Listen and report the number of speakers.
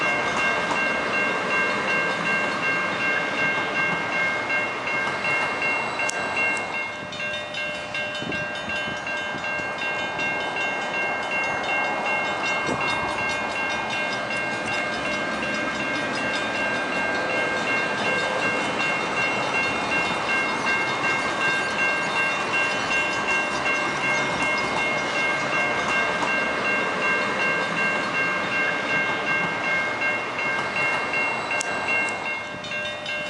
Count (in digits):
0